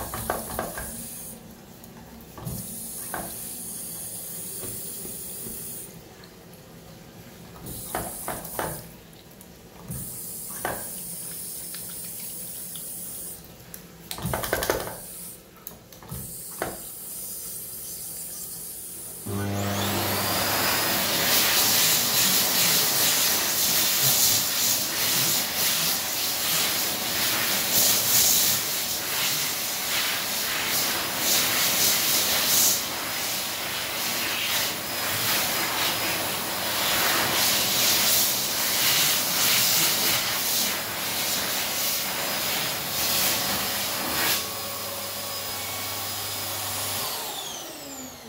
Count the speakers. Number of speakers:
zero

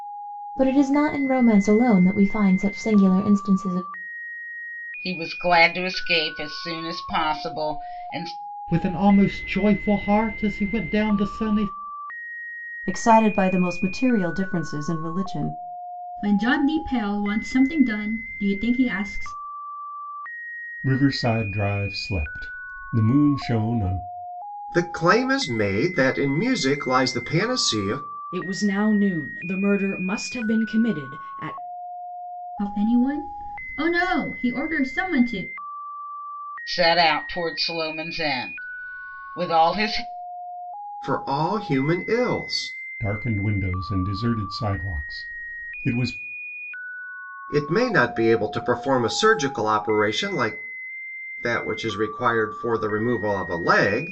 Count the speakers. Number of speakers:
eight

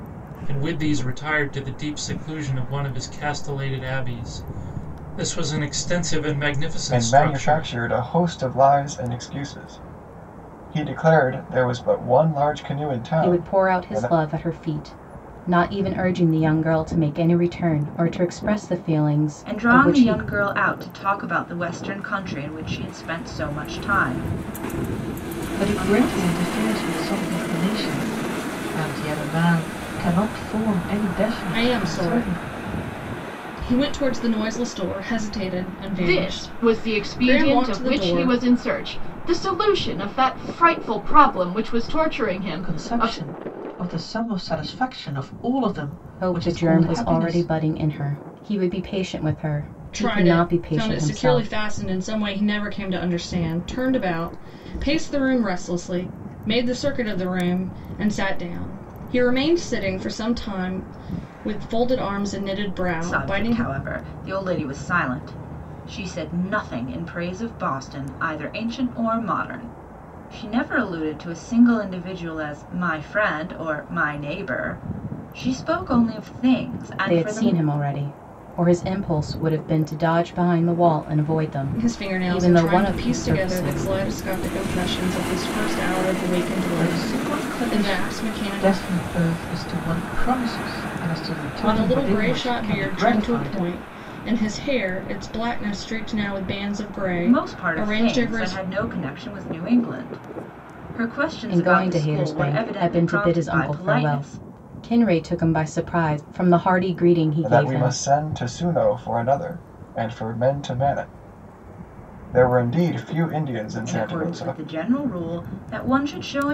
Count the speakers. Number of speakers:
seven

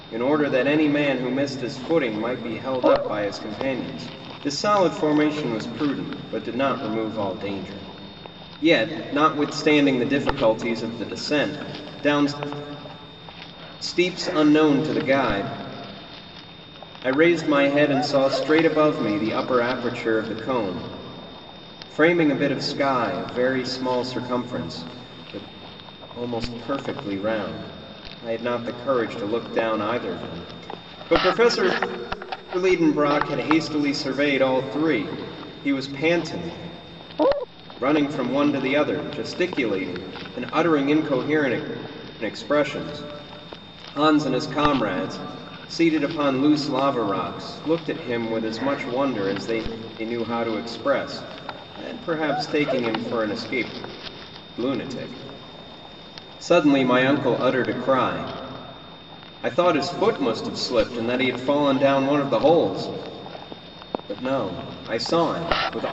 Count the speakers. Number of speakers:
one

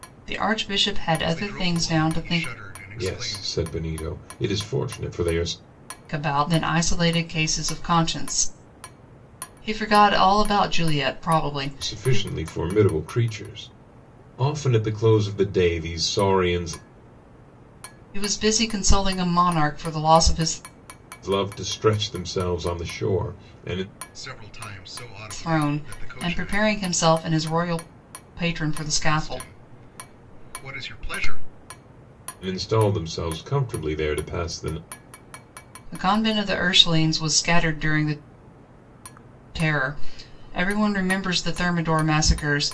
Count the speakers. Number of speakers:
three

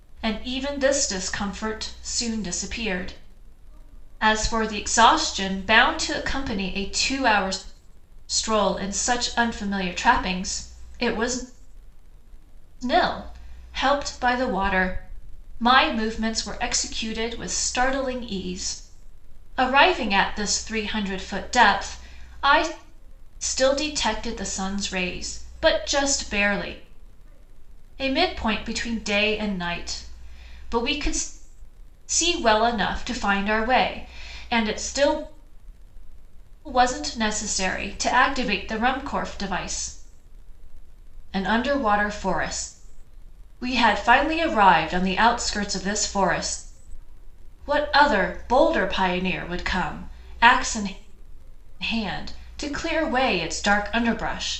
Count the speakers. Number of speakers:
one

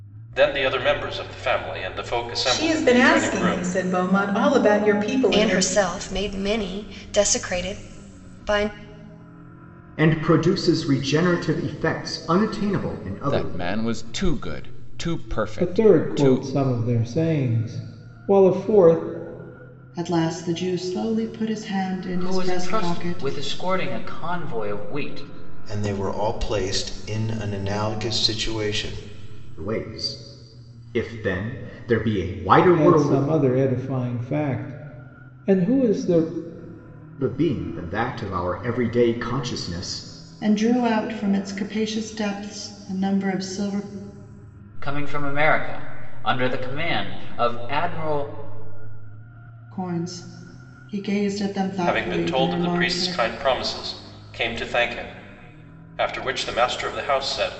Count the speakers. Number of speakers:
nine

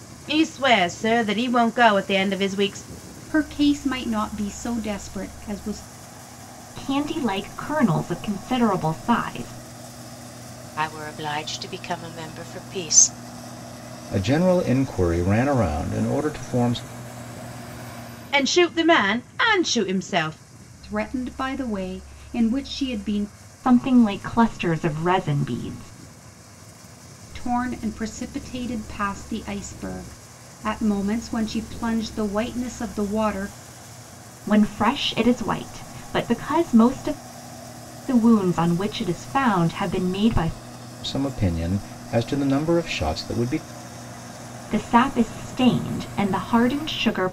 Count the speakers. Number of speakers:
five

